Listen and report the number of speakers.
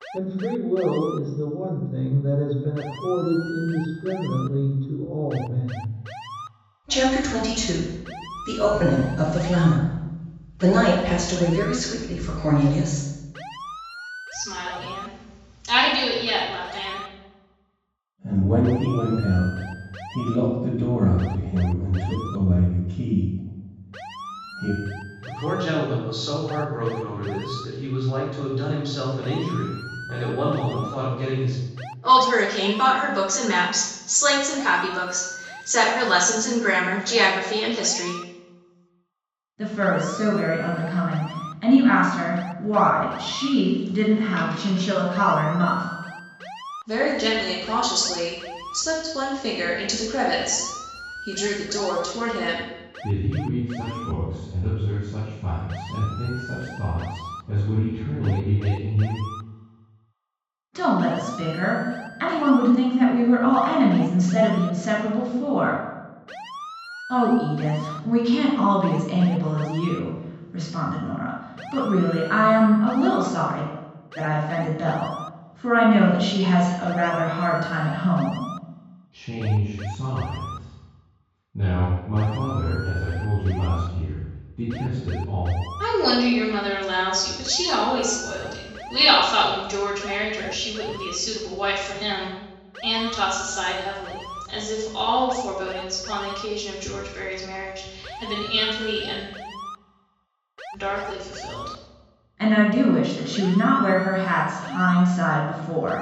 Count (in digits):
9